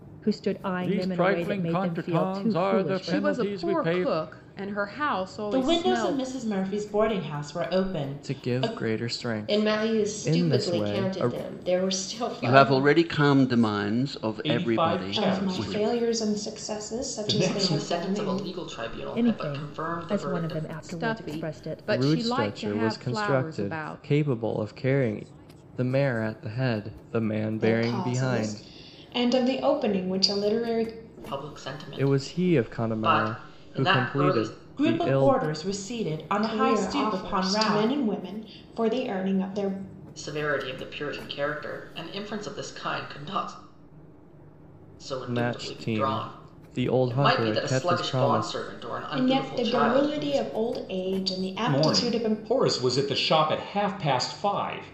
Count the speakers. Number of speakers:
10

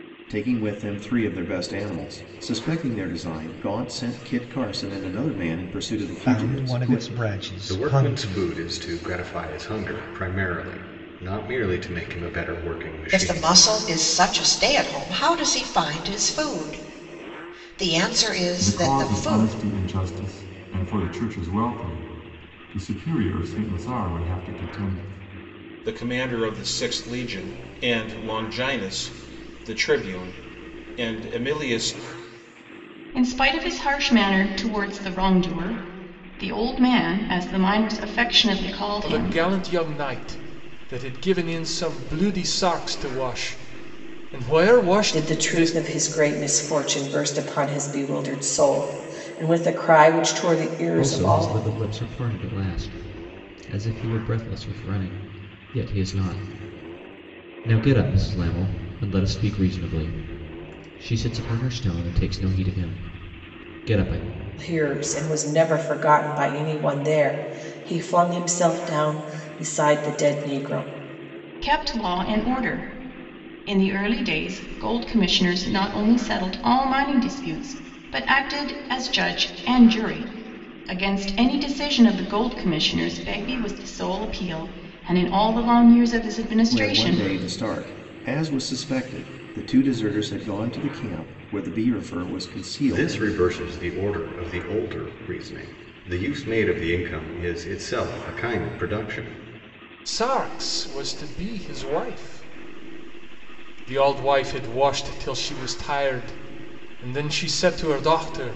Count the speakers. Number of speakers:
10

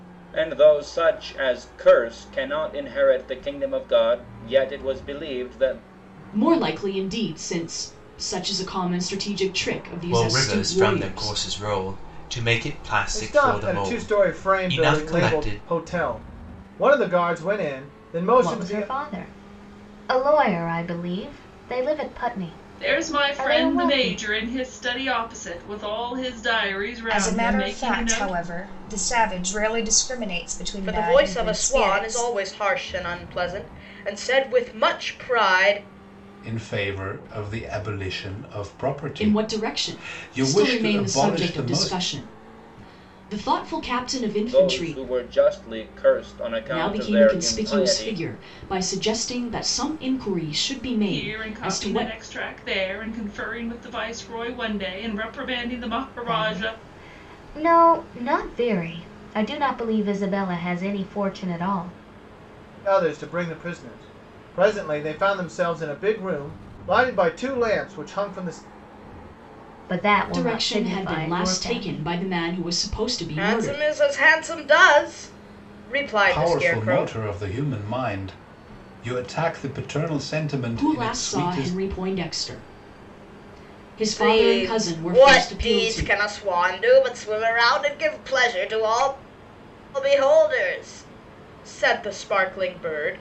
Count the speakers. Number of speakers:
9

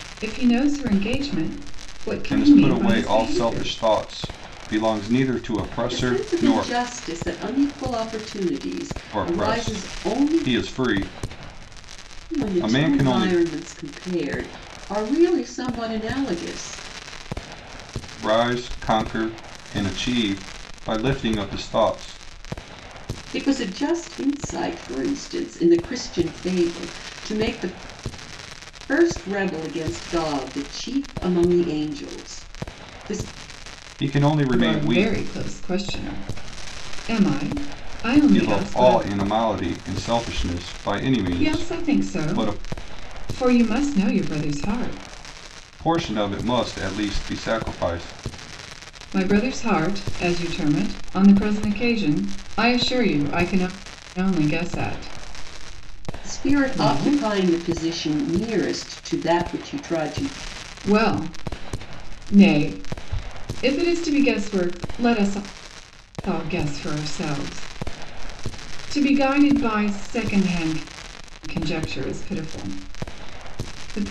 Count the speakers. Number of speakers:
3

